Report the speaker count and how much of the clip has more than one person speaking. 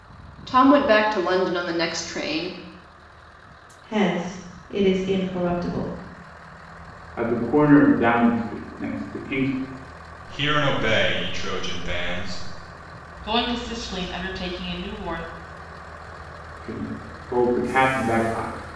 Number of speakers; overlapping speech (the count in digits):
5, no overlap